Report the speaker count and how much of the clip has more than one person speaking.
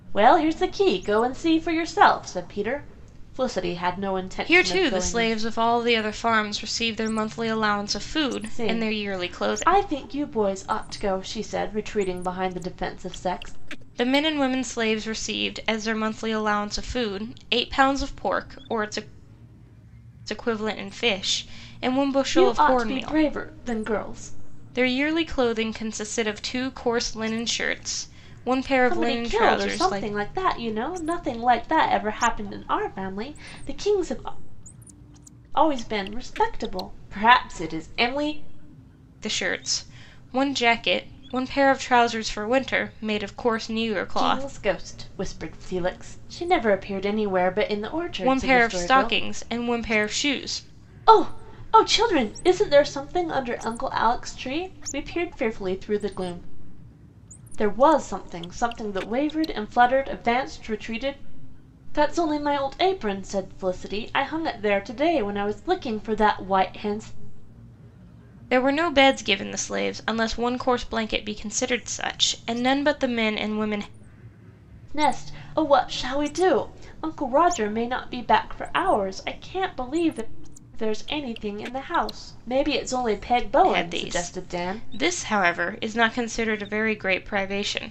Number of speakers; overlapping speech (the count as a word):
two, about 8%